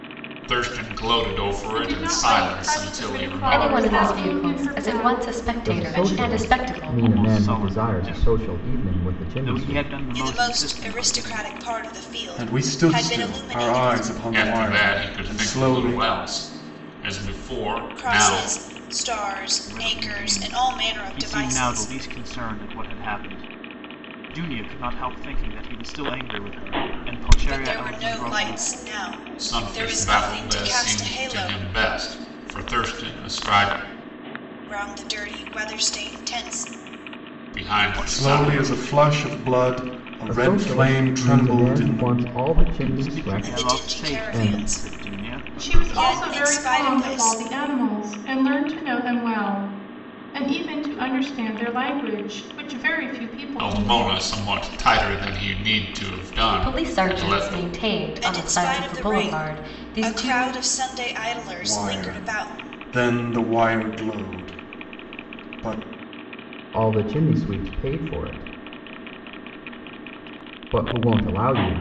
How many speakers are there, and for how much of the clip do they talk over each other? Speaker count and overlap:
seven, about 45%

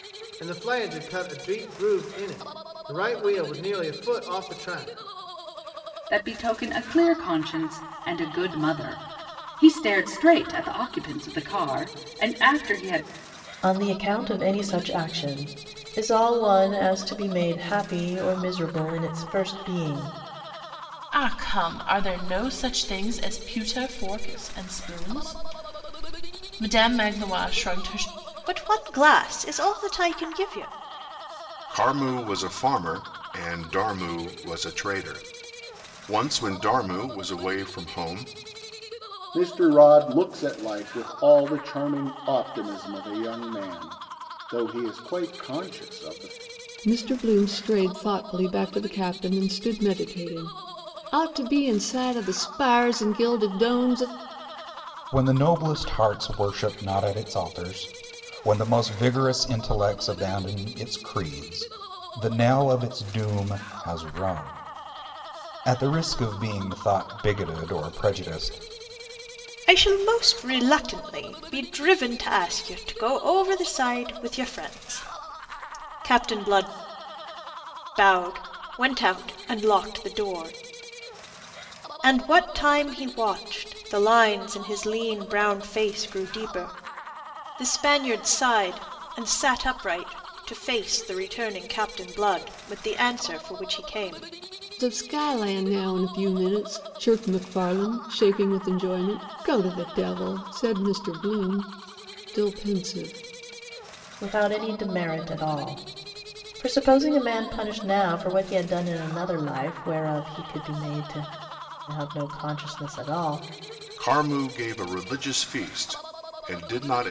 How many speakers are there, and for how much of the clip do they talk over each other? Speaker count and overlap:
nine, no overlap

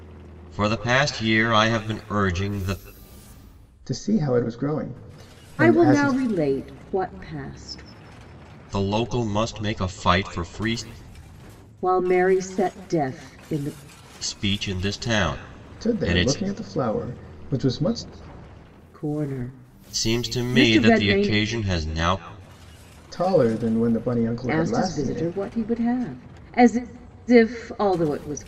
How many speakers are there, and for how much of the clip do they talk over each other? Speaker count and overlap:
three, about 13%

